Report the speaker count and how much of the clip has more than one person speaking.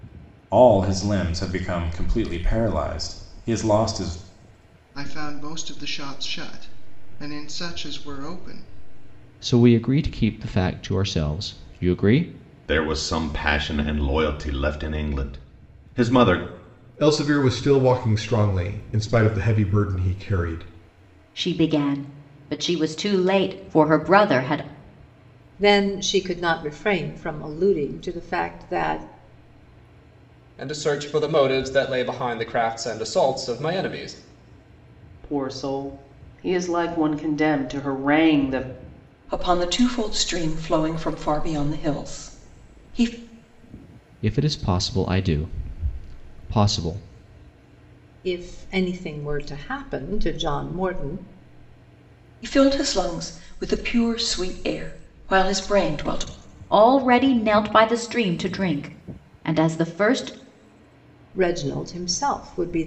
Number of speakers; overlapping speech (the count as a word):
ten, no overlap